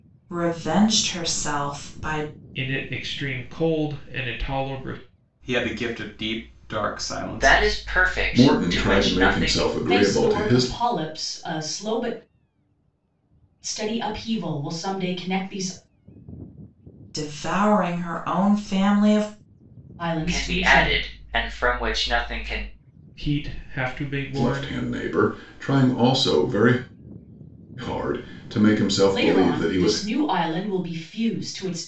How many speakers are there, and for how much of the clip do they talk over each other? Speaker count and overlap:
six, about 15%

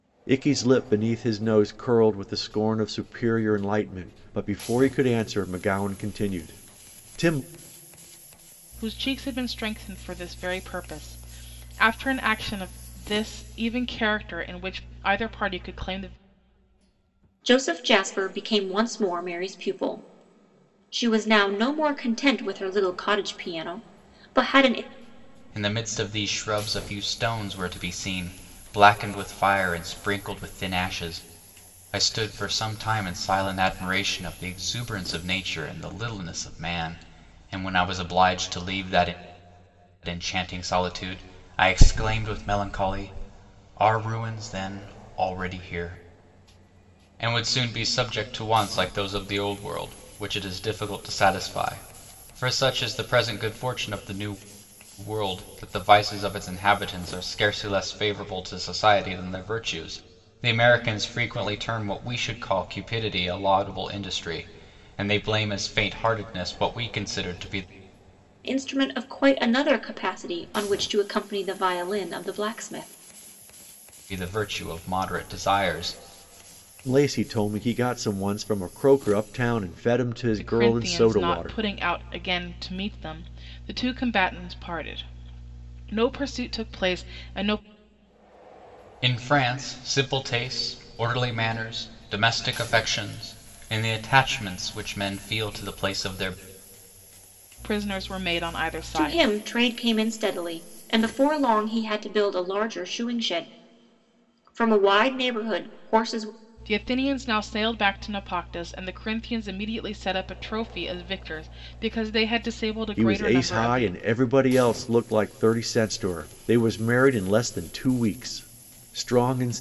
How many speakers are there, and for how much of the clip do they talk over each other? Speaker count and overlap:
four, about 2%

